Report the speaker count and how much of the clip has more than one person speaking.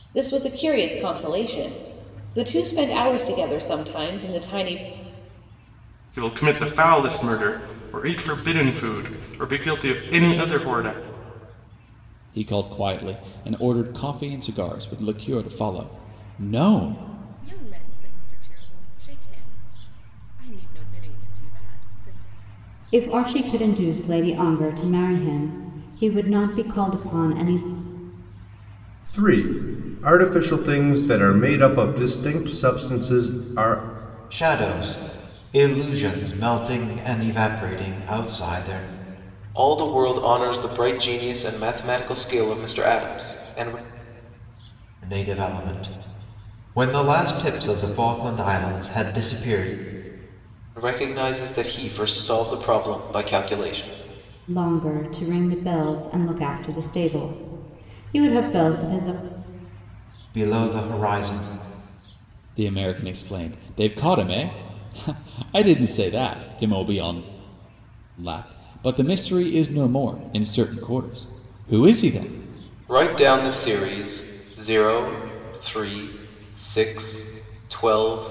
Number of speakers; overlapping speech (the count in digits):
8, no overlap